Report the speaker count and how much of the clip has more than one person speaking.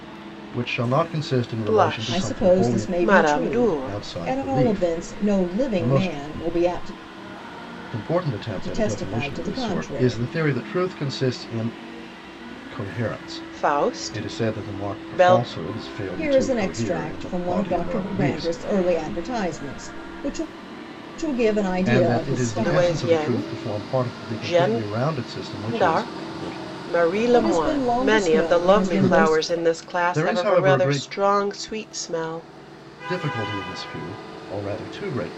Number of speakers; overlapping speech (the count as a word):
three, about 52%